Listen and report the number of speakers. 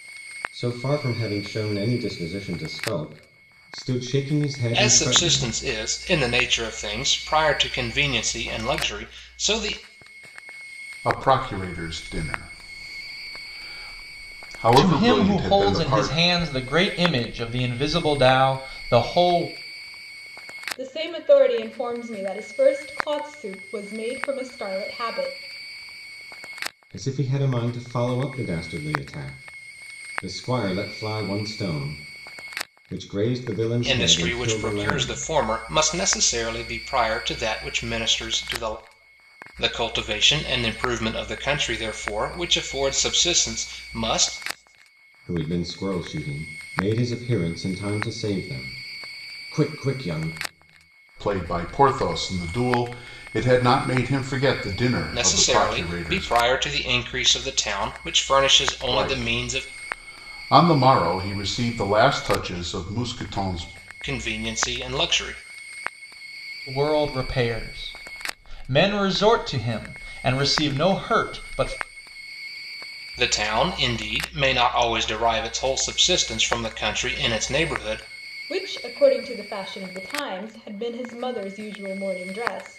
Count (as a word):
five